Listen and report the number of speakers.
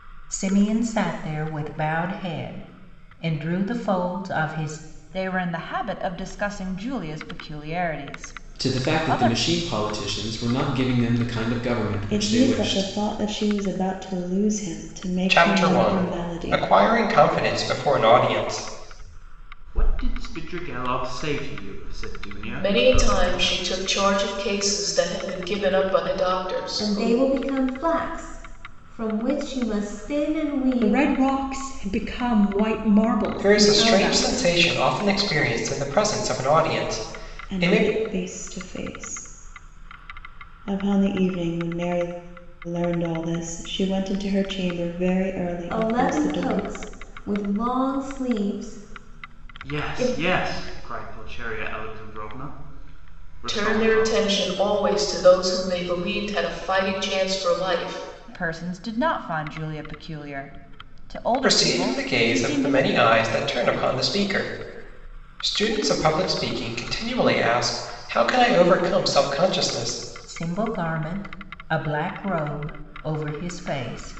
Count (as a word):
nine